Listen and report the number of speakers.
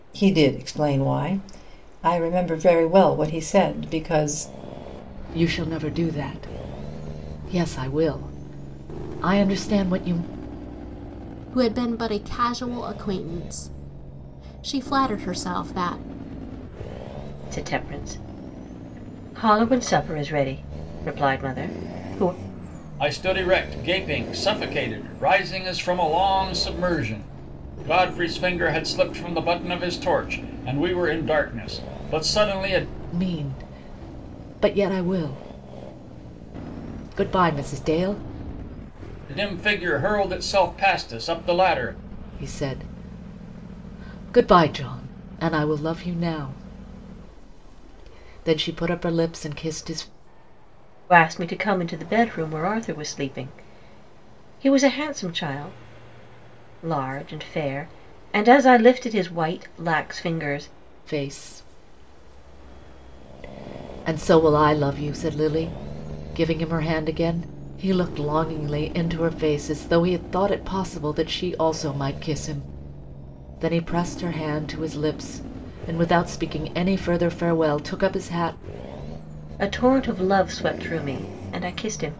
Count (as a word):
five